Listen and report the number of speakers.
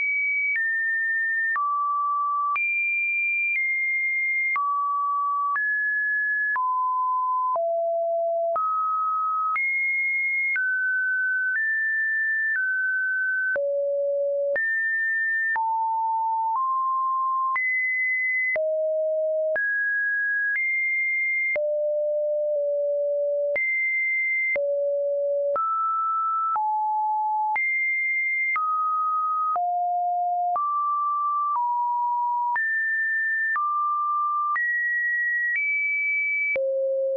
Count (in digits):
0